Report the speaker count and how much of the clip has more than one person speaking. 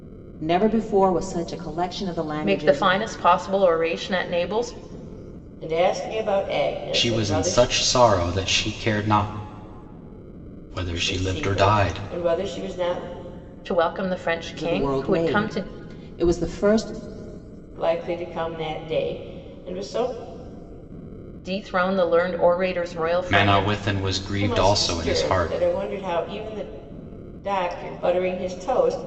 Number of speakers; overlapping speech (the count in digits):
4, about 18%